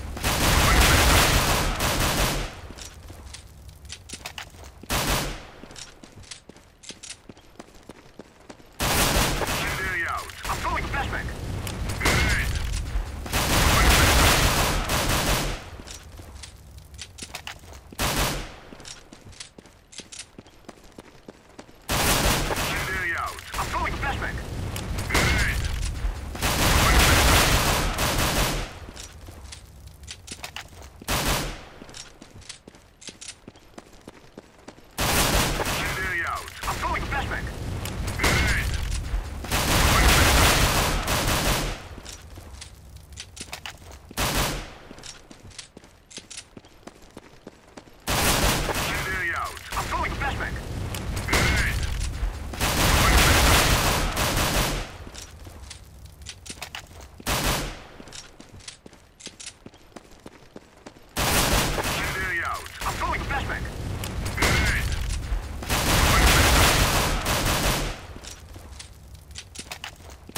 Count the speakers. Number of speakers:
0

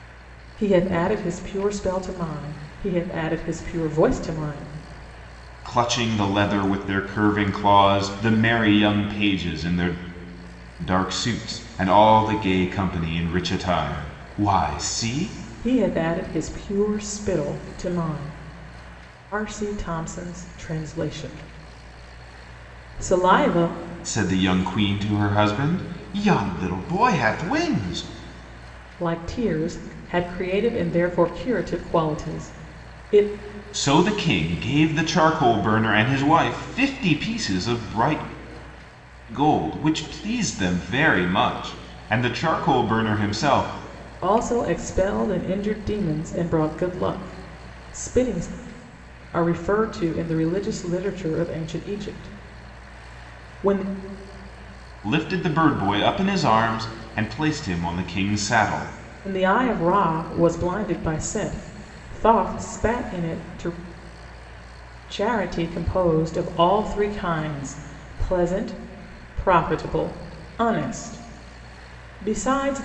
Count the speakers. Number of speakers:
2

